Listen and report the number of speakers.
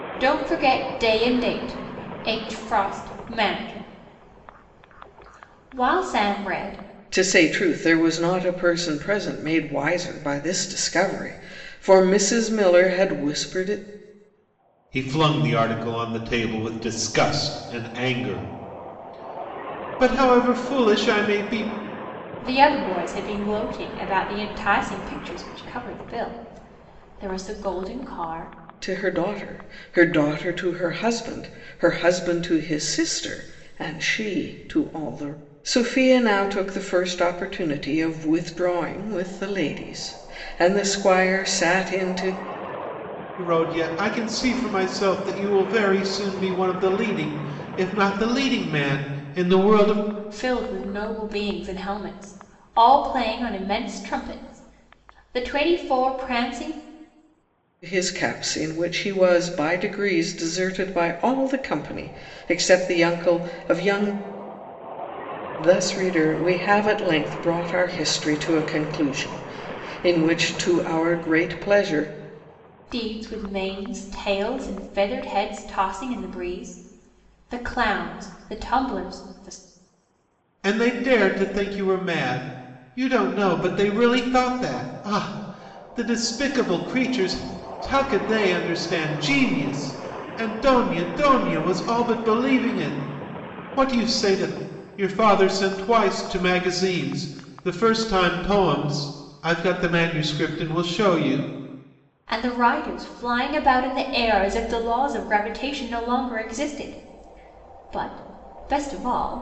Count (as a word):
three